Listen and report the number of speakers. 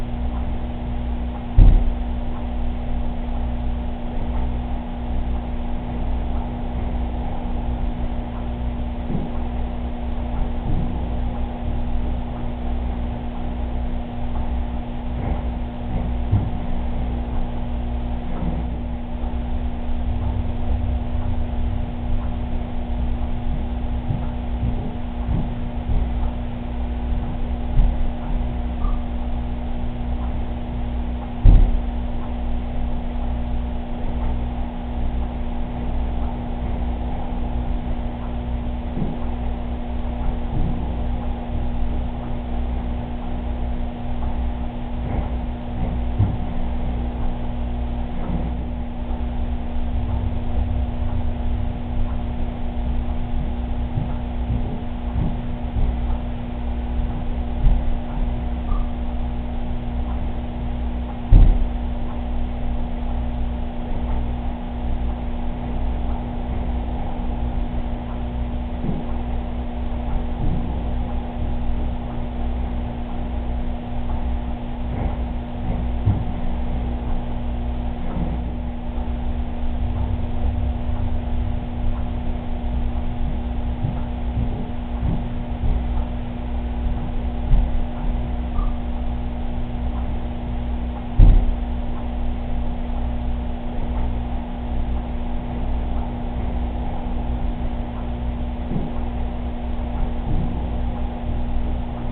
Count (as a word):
zero